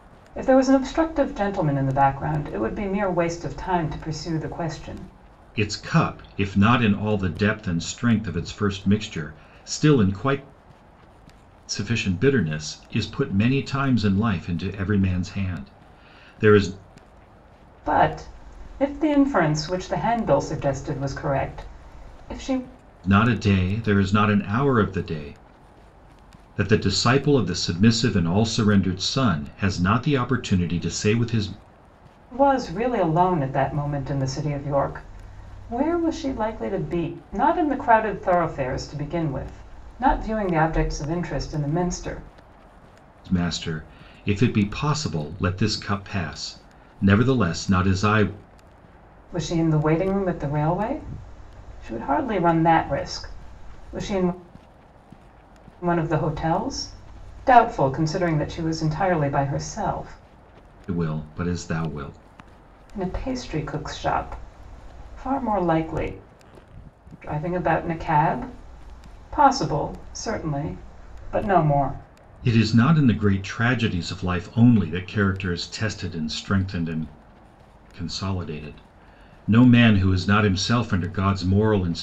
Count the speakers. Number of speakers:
two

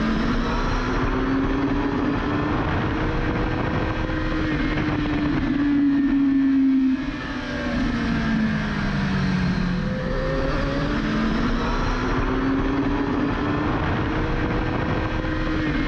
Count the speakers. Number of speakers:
zero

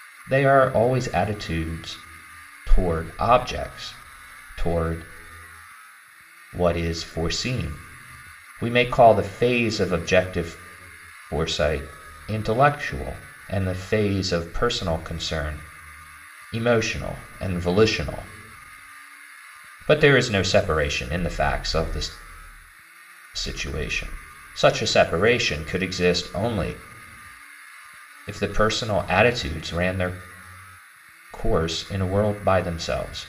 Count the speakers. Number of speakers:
one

